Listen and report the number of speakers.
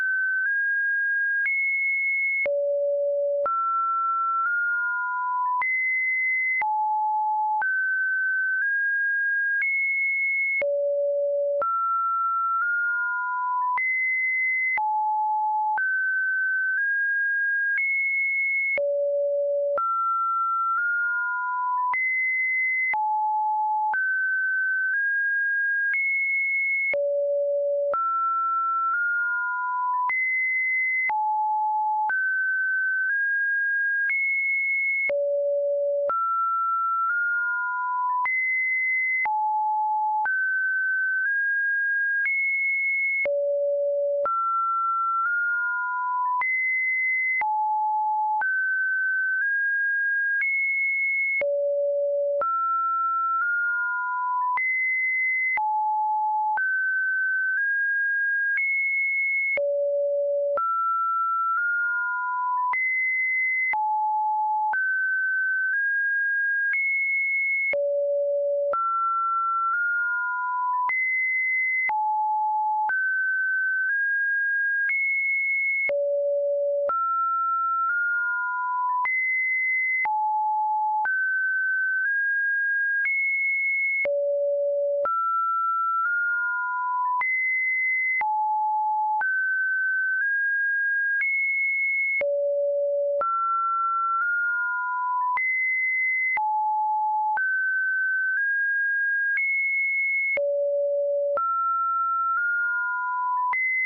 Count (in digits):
0